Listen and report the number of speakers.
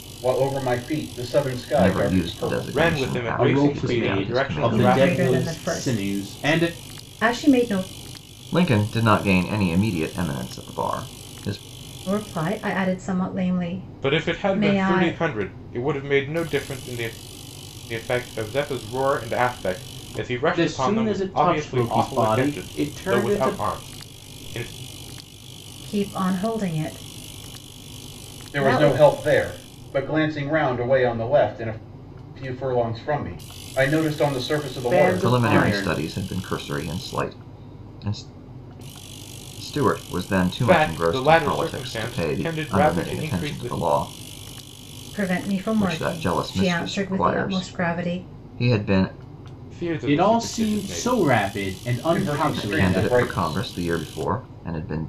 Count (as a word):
five